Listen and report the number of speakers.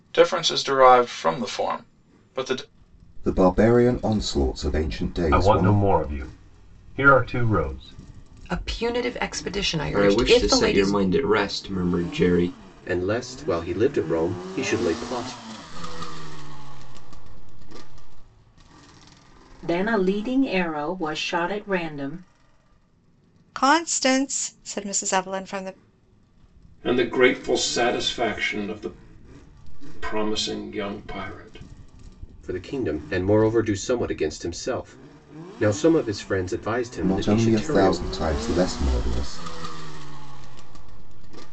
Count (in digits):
10